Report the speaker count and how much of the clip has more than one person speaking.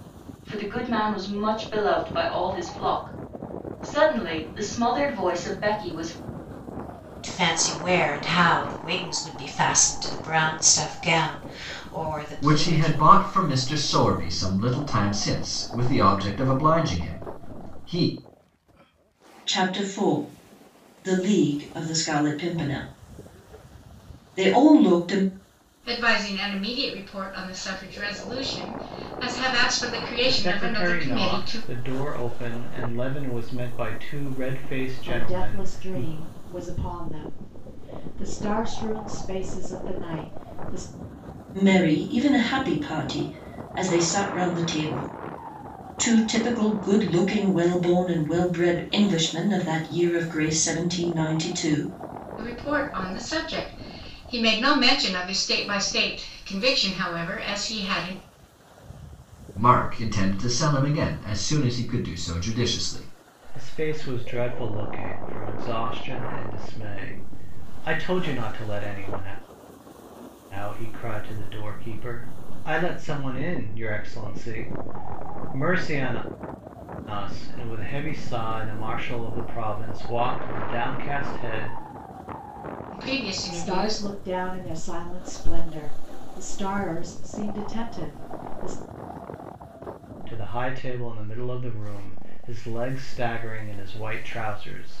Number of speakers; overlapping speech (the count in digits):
7, about 4%